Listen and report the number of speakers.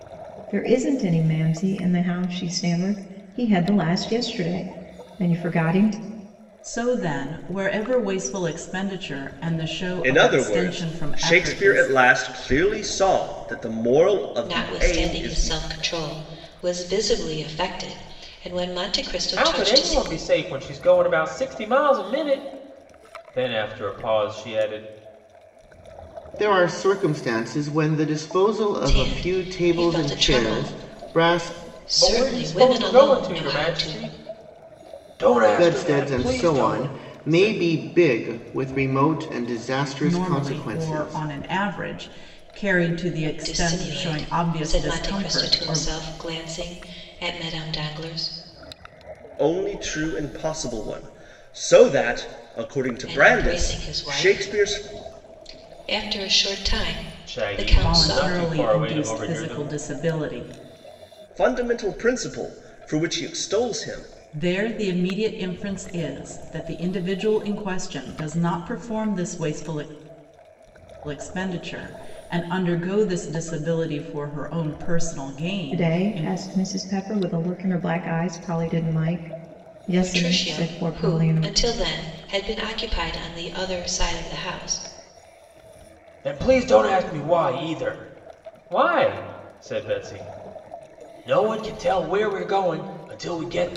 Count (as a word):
six